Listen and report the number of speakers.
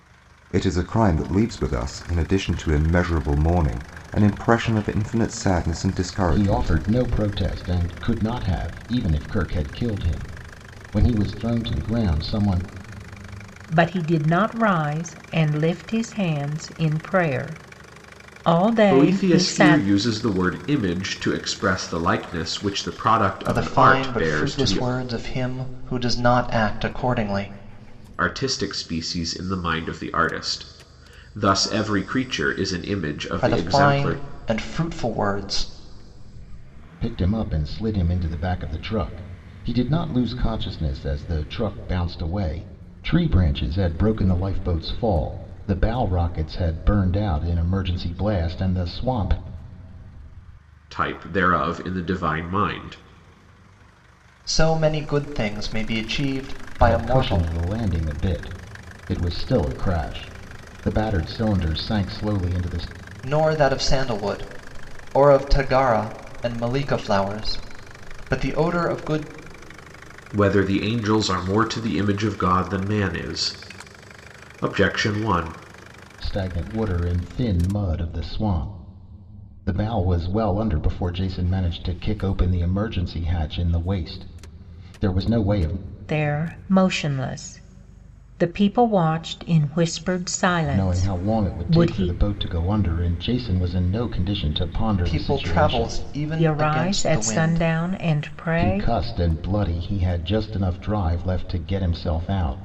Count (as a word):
five